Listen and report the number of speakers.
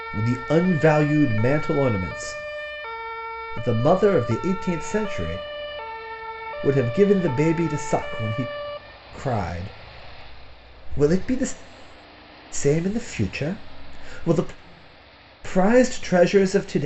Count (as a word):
one